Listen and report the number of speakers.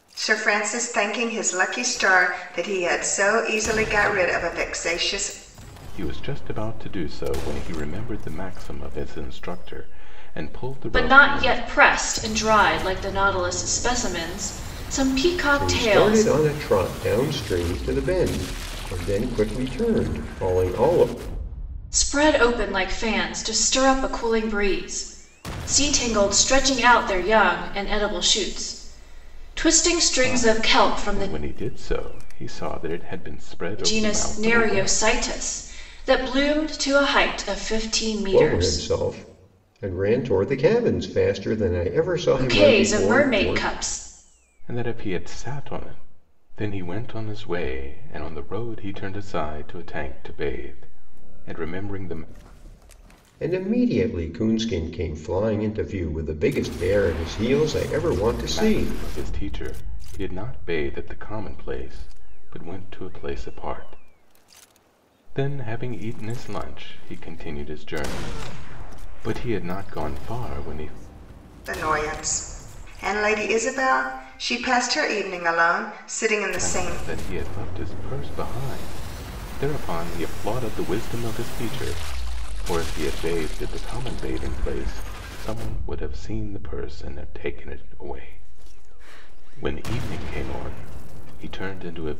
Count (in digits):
4